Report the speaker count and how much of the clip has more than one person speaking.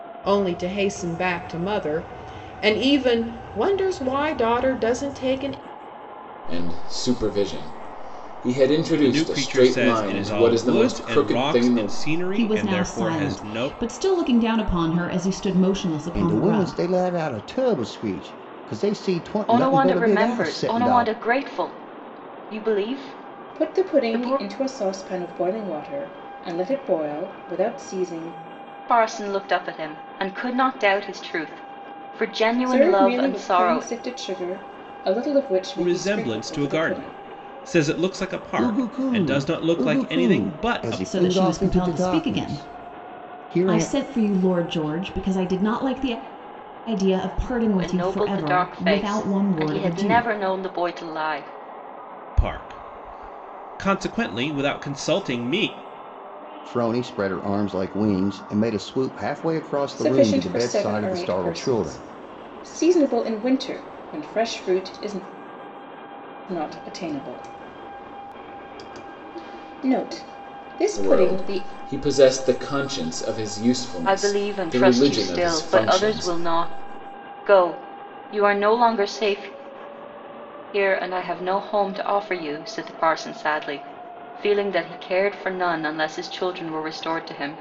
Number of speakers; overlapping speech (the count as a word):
seven, about 27%